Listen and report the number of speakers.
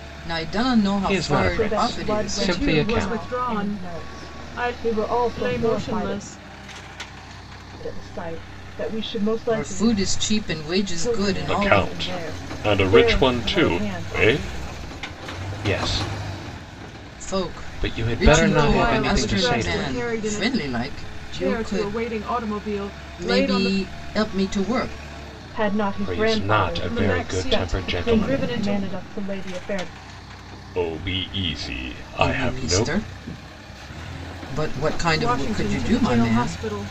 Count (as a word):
four